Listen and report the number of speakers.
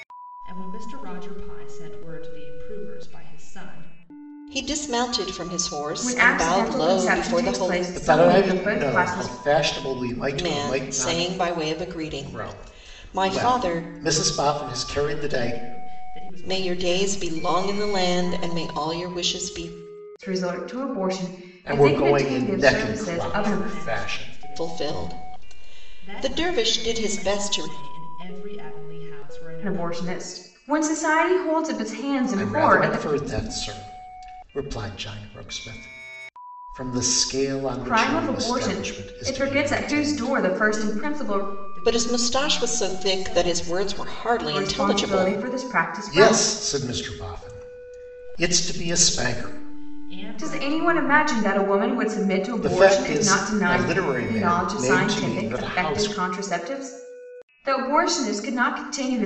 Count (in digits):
4